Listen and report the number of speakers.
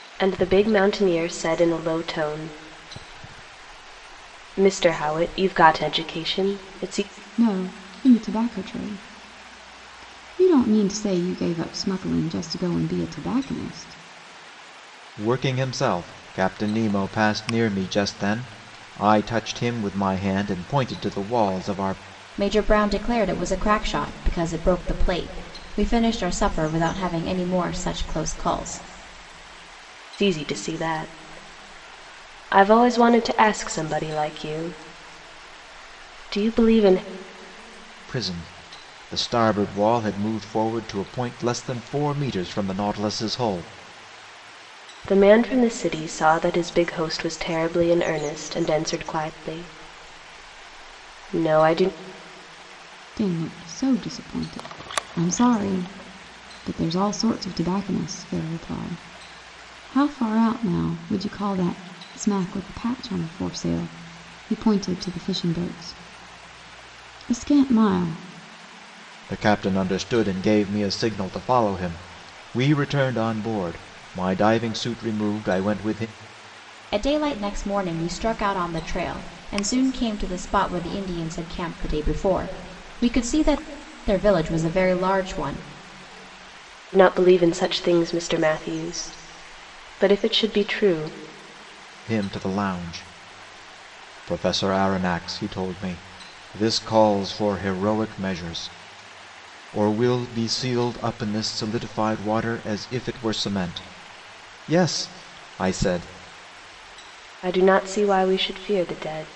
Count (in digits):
4